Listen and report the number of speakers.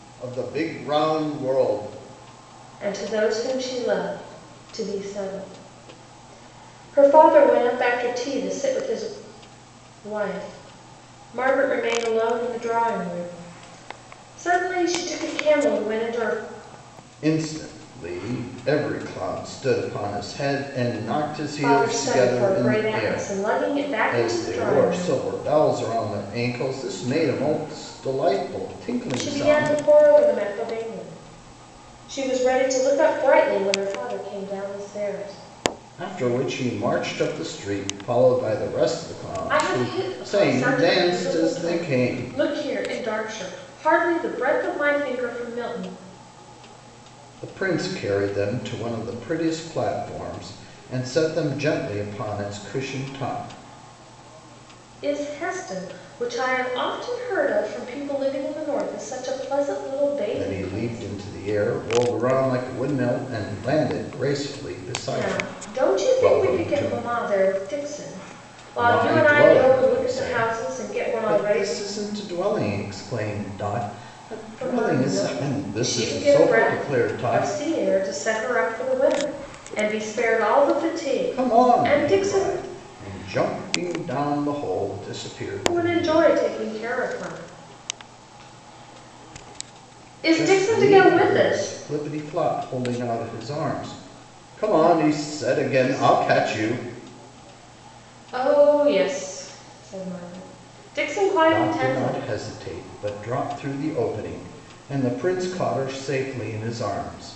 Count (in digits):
2